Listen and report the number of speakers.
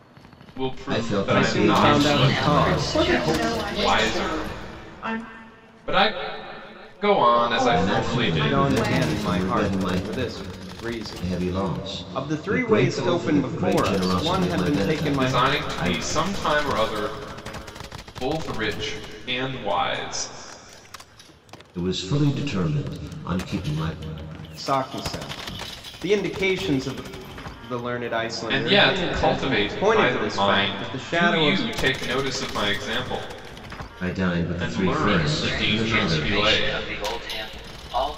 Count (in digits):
6